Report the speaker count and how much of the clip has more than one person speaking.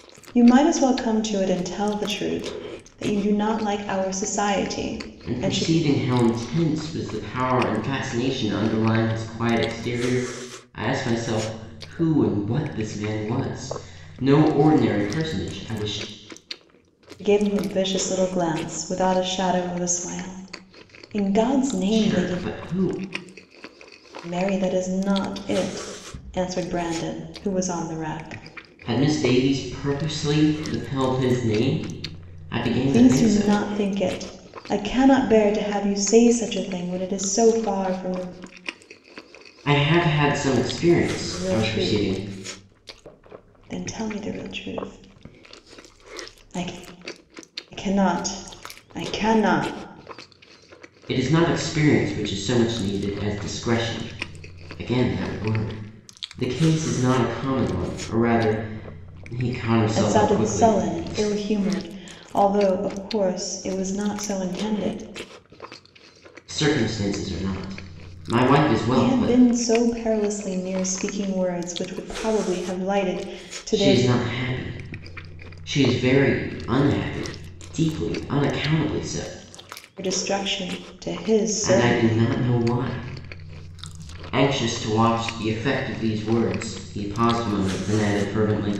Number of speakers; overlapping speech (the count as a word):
two, about 6%